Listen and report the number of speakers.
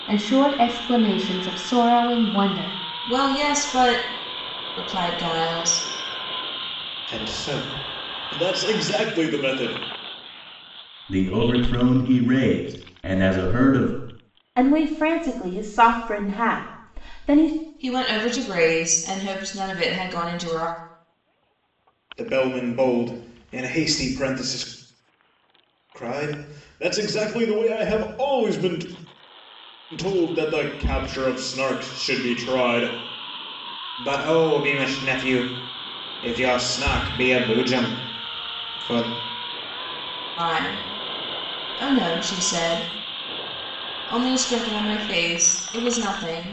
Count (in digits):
5